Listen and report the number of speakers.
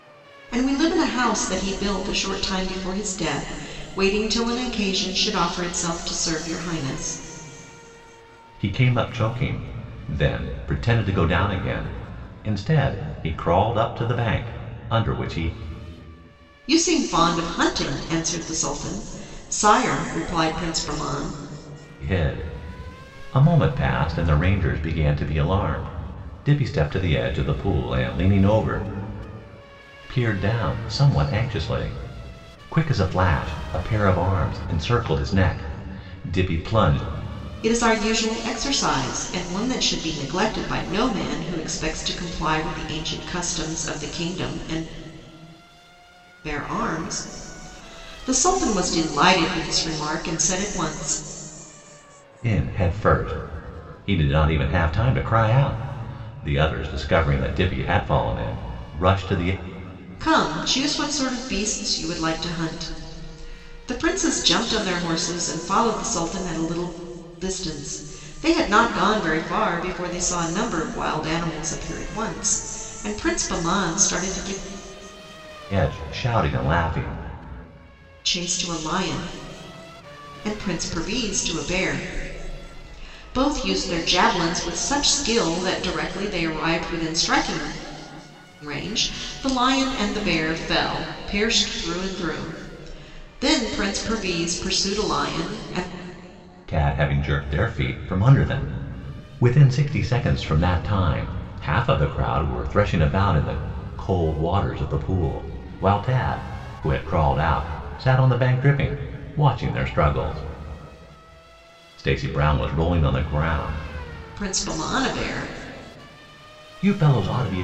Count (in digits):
2